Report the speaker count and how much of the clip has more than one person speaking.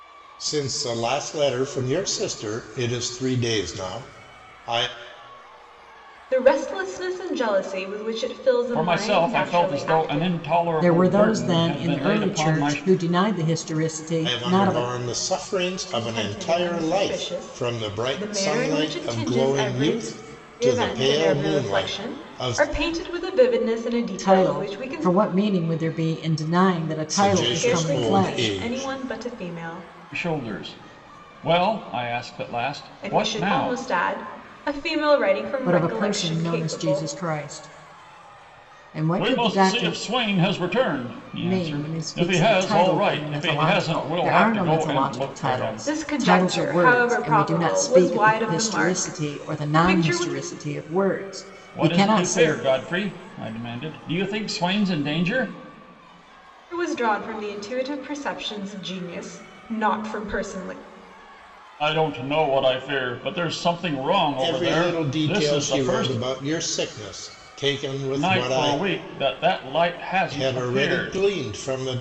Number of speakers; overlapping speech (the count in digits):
4, about 41%